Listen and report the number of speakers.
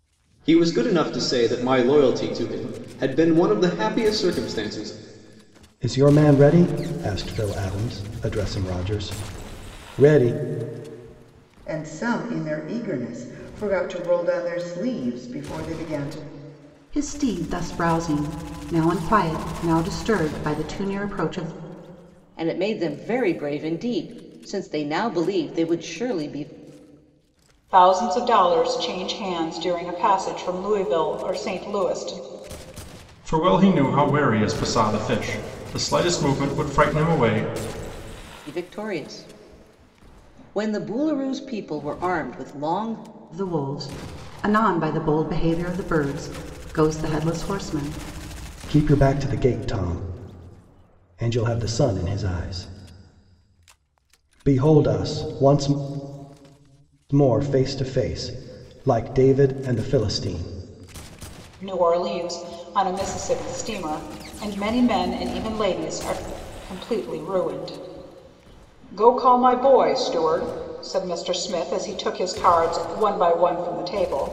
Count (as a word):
seven